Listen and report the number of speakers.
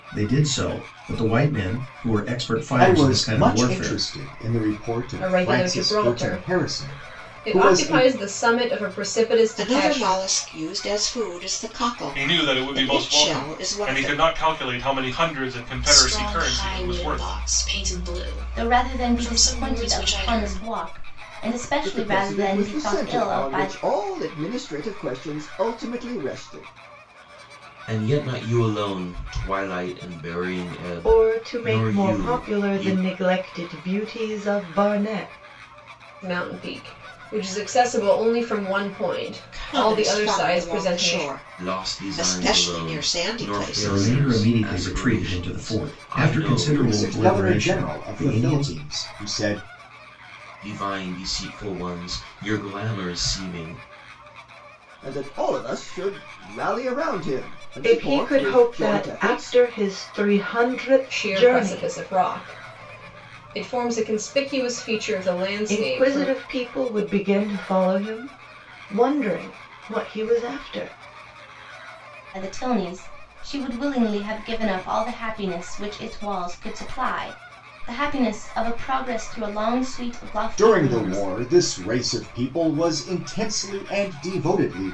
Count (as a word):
ten